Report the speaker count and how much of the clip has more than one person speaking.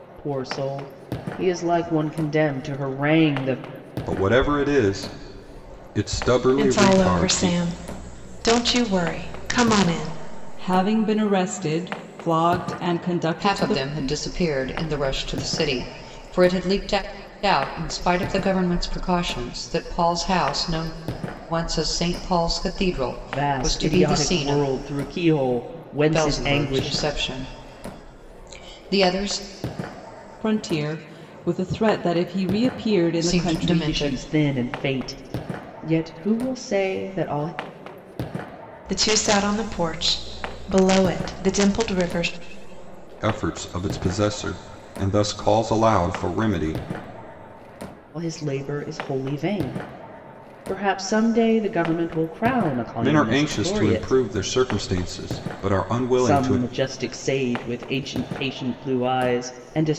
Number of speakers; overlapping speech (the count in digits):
5, about 11%